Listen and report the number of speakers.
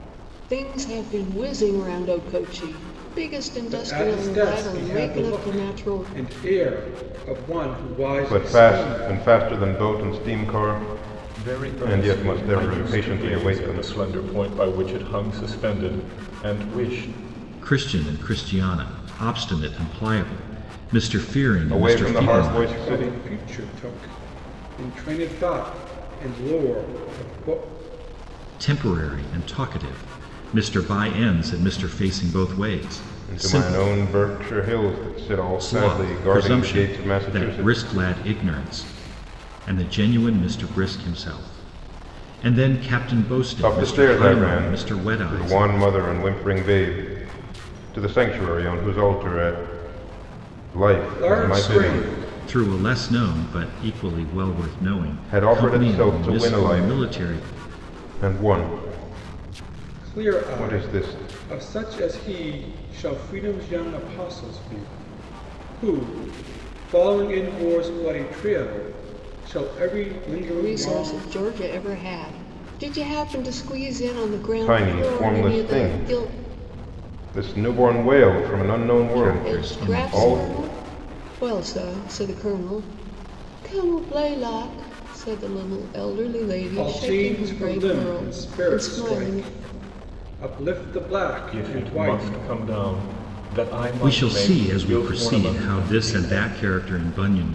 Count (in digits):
5